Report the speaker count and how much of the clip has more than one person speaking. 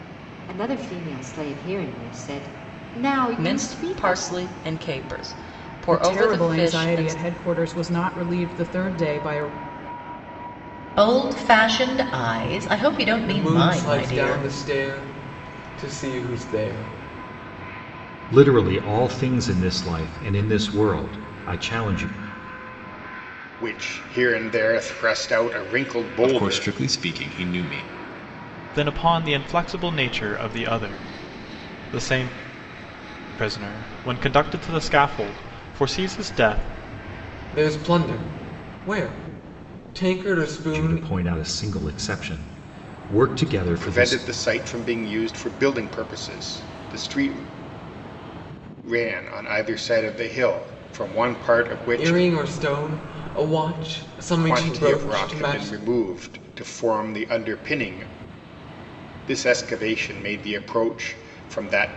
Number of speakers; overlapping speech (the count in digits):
9, about 11%